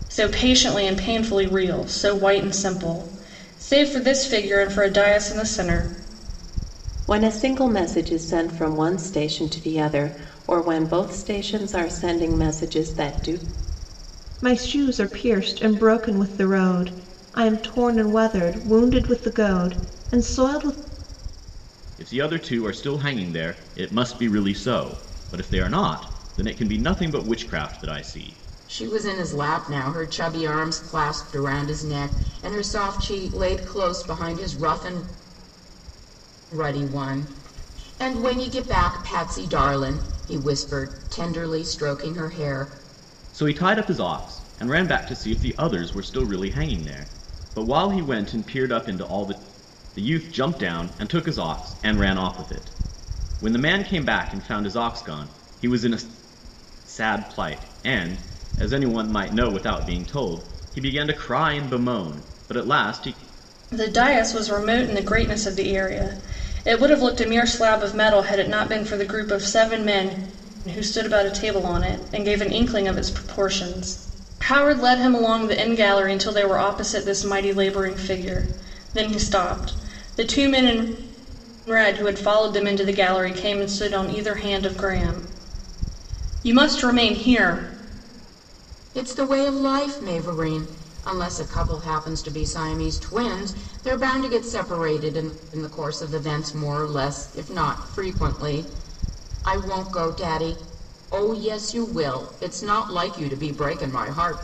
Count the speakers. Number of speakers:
5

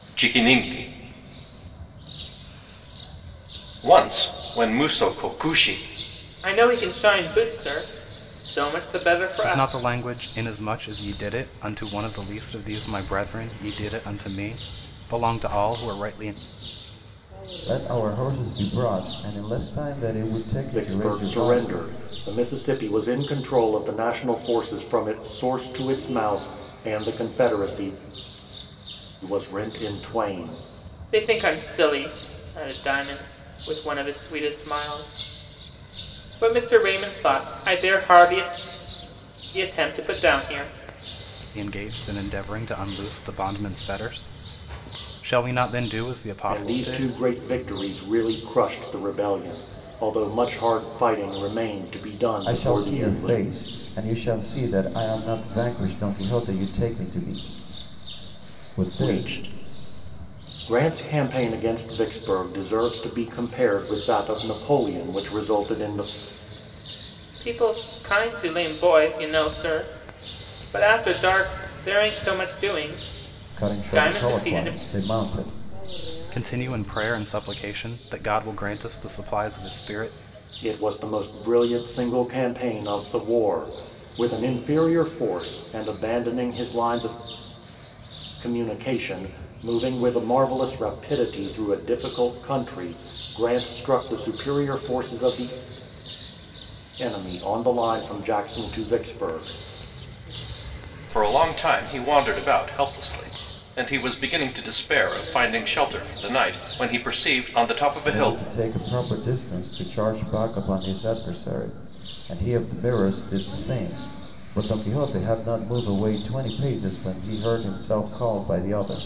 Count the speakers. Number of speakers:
5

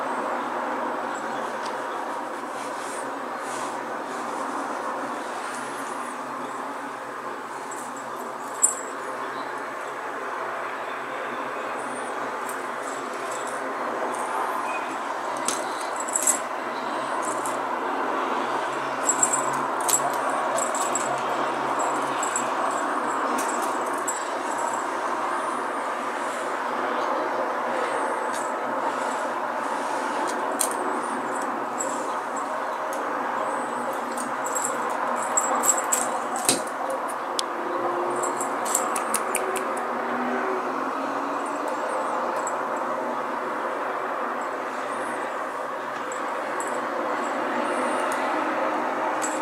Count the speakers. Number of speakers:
0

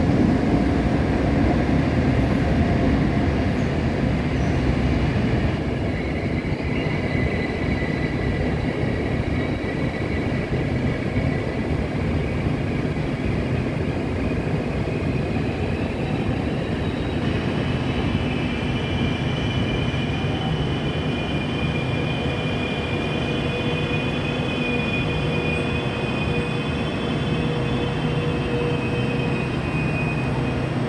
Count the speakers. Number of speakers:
0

